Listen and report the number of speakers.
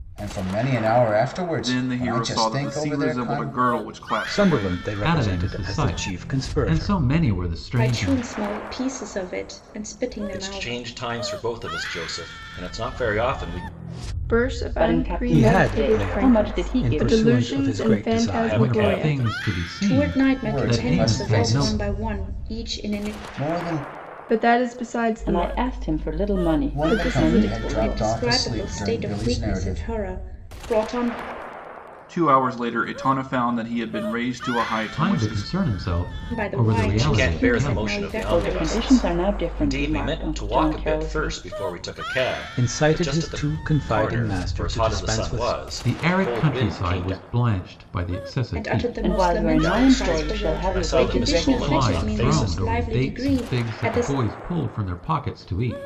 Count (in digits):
8